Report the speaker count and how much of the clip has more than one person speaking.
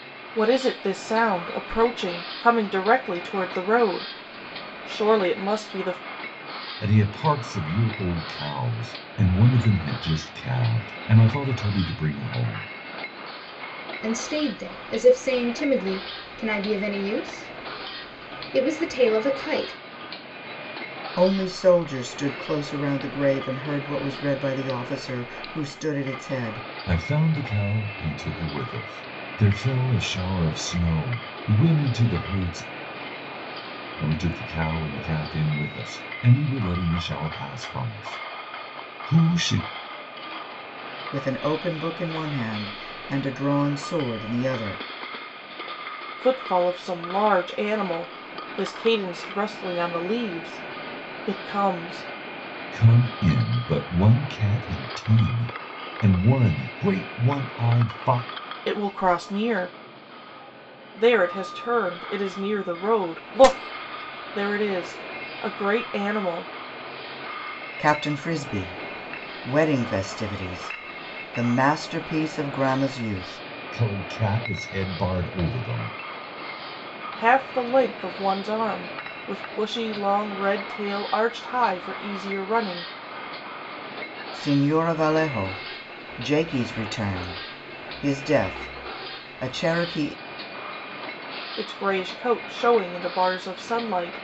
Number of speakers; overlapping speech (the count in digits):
4, no overlap